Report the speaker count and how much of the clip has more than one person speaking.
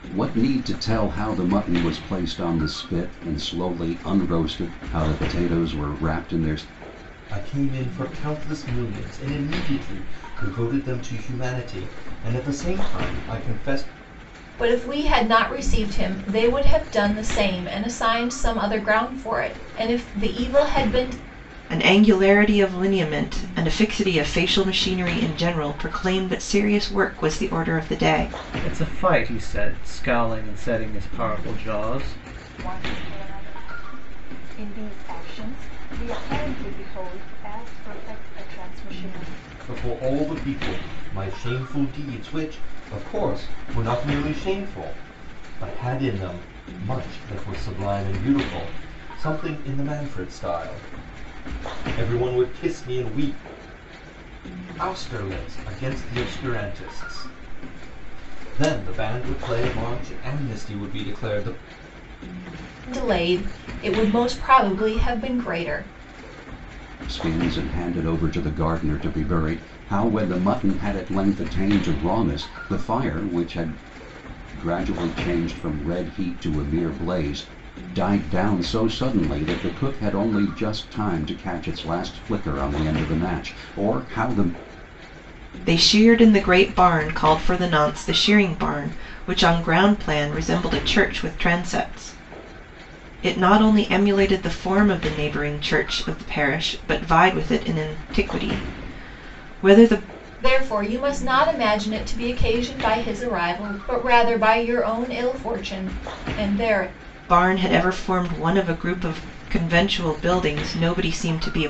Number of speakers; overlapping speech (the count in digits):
6, no overlap